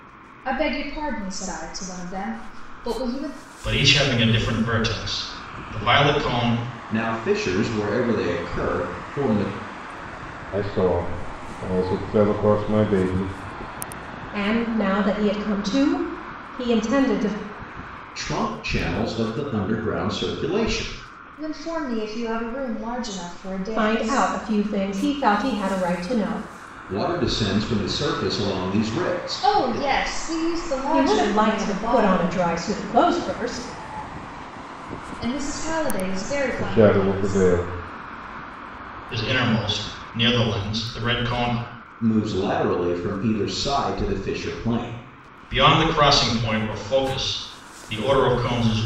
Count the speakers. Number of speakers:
five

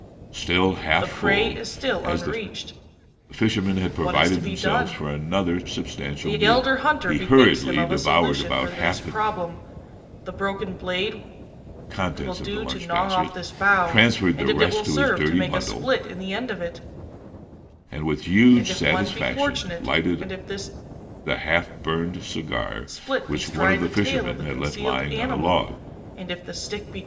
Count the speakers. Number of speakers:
two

